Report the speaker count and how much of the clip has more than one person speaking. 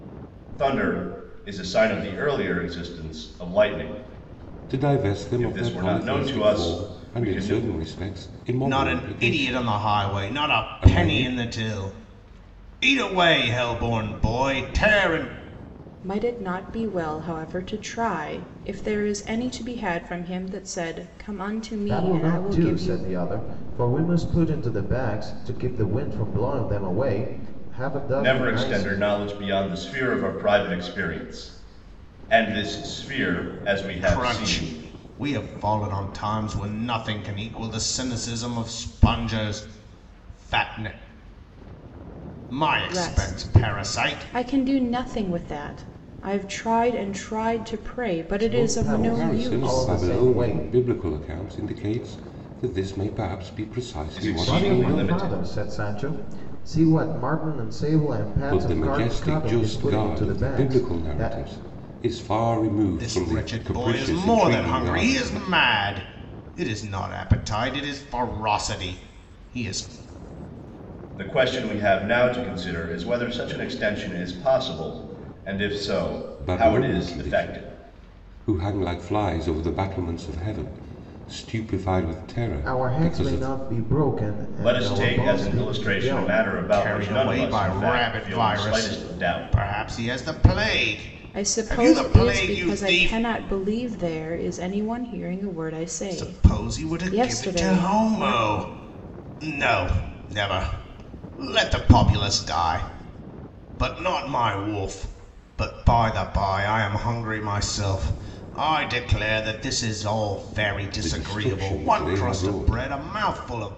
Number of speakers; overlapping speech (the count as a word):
five, about 28%